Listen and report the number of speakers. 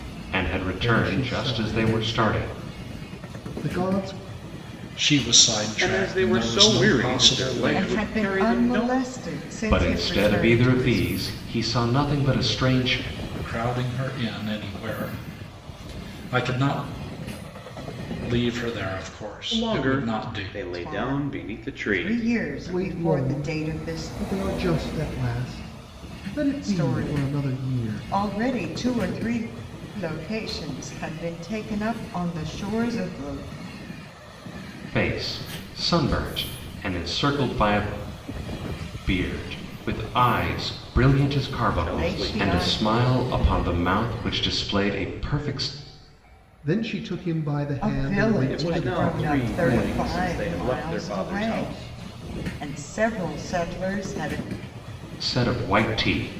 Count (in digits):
5